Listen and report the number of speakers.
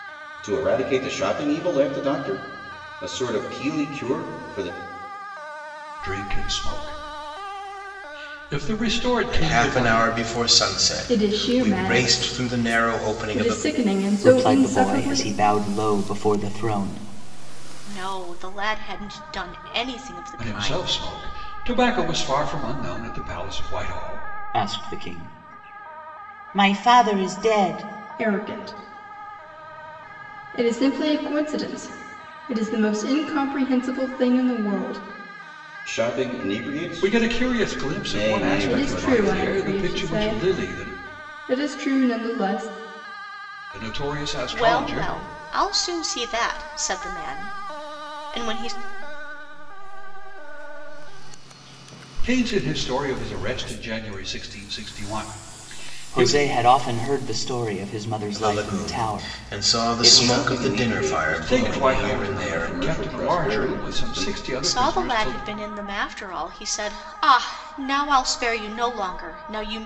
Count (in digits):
7